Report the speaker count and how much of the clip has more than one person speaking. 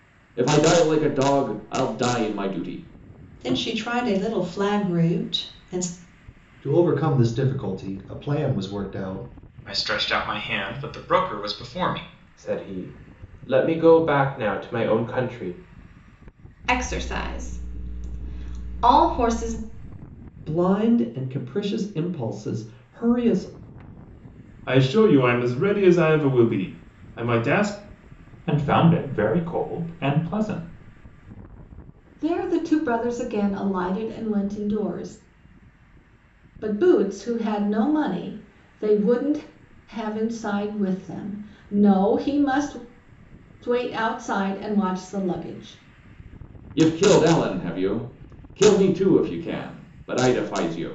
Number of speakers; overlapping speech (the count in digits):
10, no overlap